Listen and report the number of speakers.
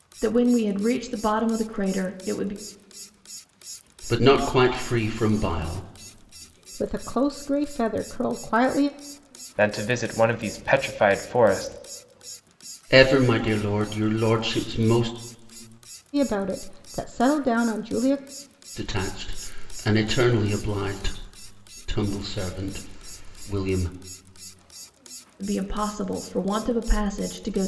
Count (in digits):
4